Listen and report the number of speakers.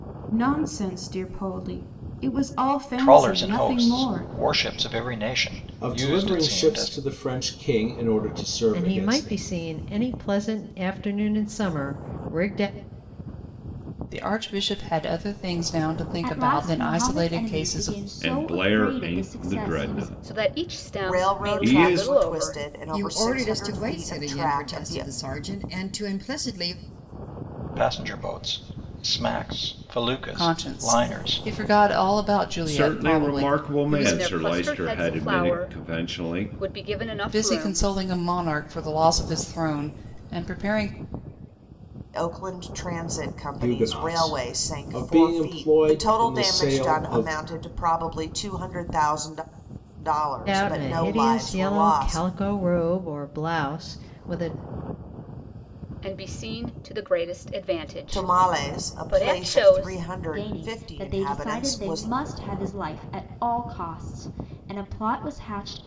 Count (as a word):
ten